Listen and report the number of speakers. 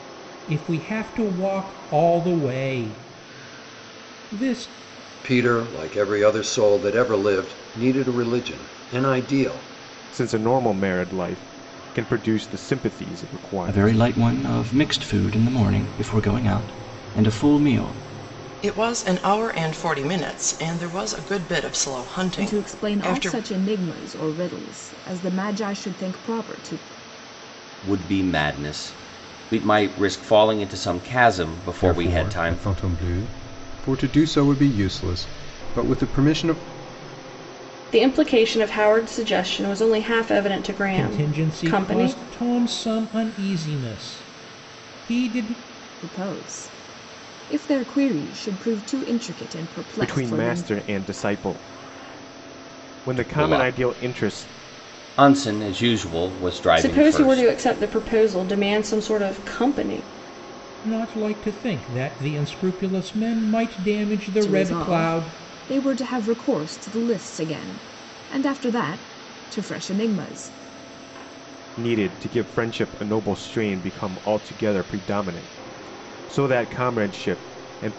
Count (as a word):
nine